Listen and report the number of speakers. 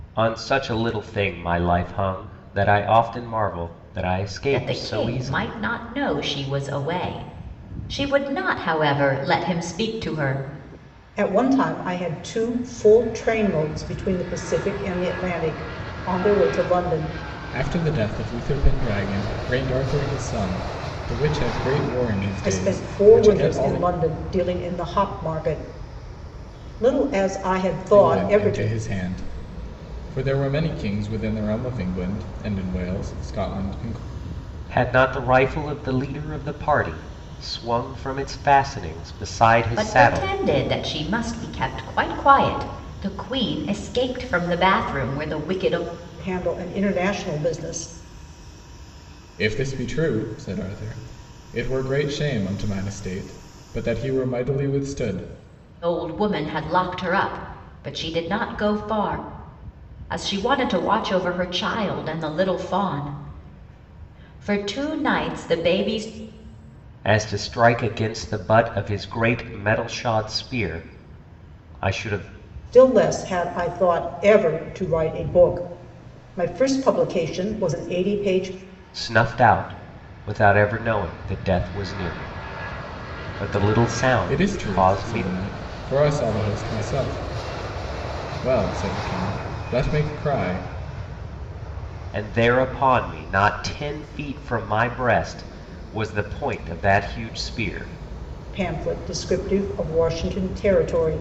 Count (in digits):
4